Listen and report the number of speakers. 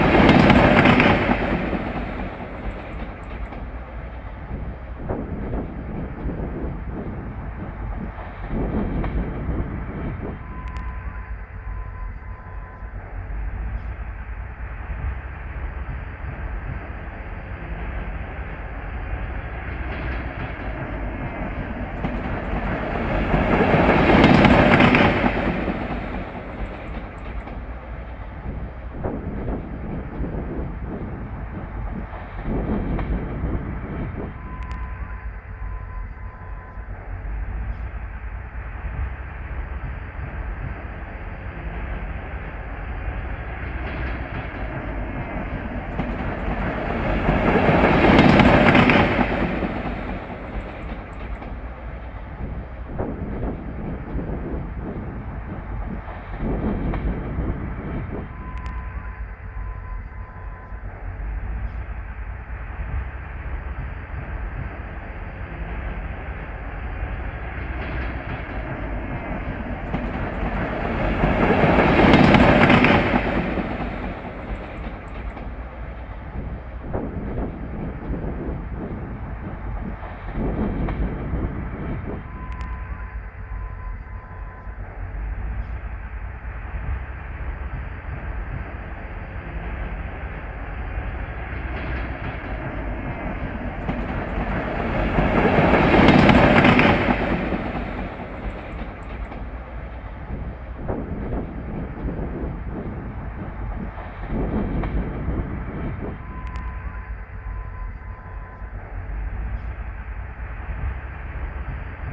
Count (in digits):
0